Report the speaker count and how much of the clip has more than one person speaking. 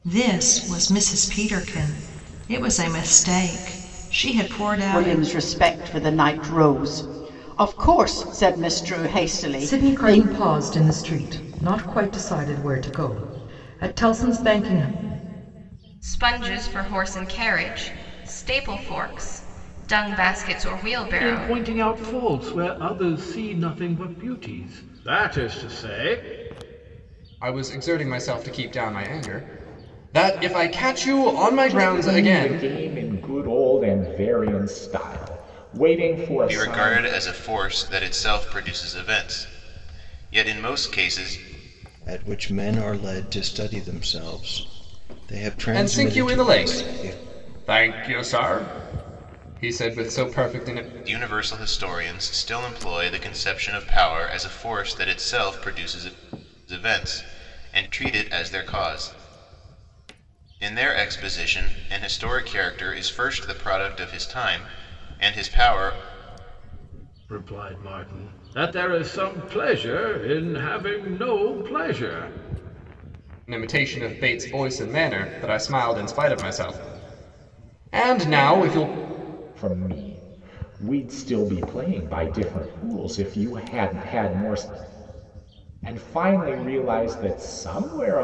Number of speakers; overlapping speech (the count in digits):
9, about 5%